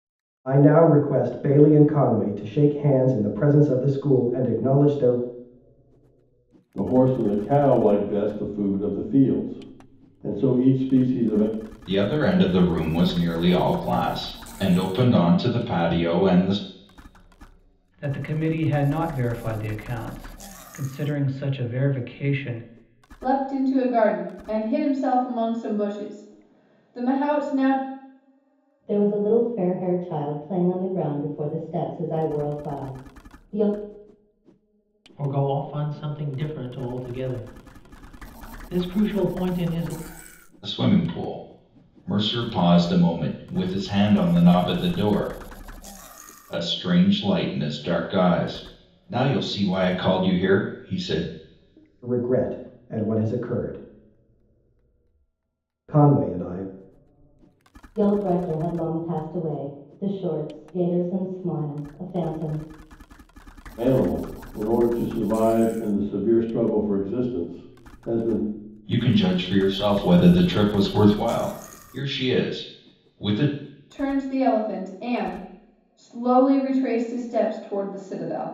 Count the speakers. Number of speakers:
seven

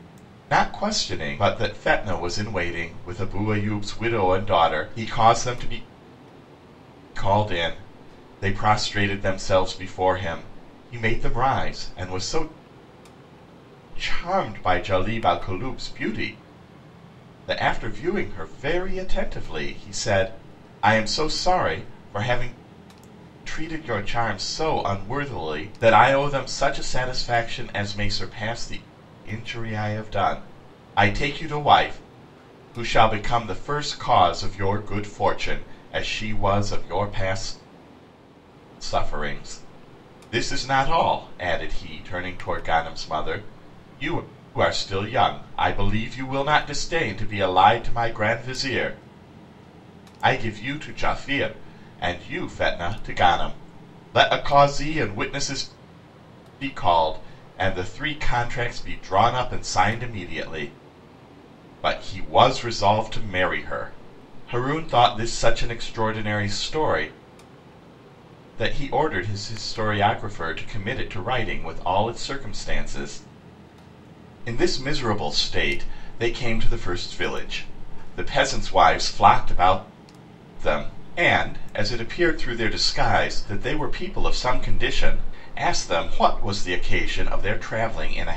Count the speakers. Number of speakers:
one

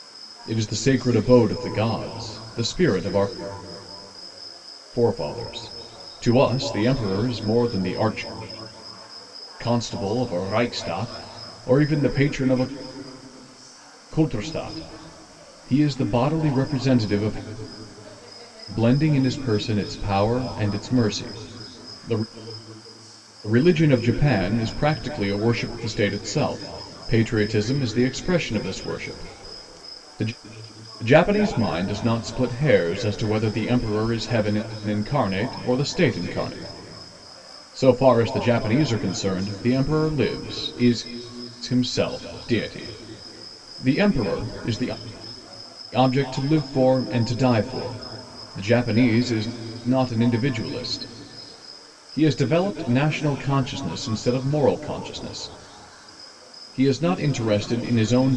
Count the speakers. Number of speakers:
one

